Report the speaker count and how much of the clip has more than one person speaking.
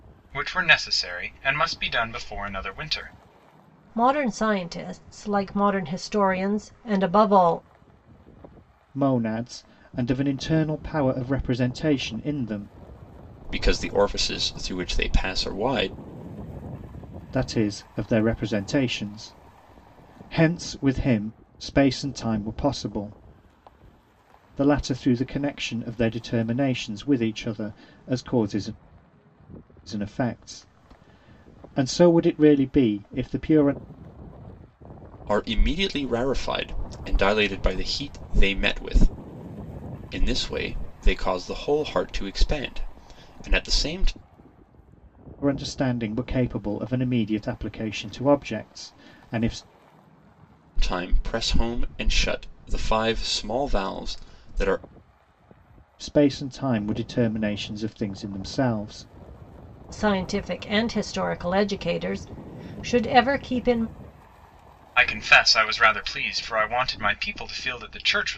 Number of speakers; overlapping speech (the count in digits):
4, no overlap